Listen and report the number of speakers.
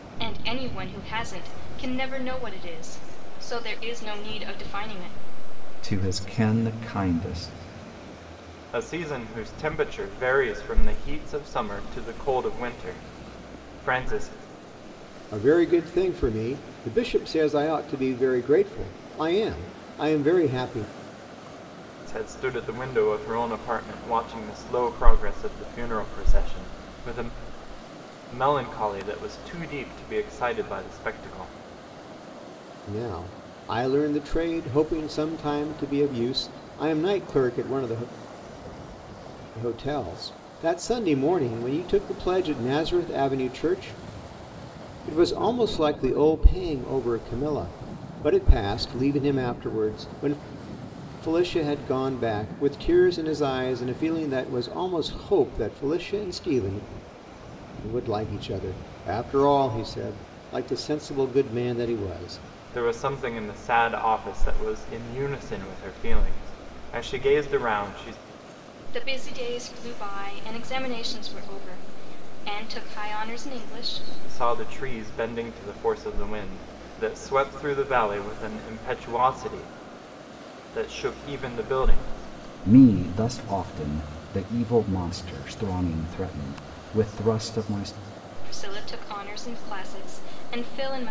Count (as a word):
four